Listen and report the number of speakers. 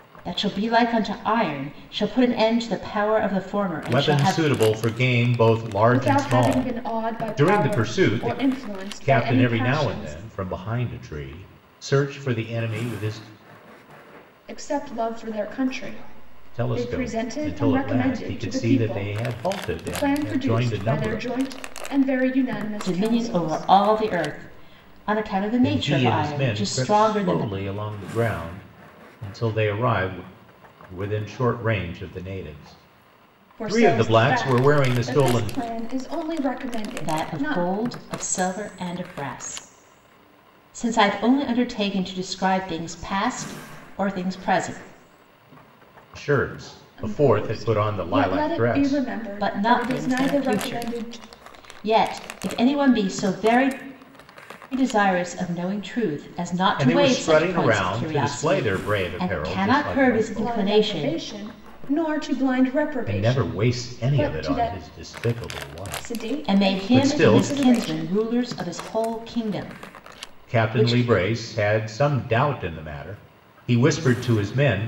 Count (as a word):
three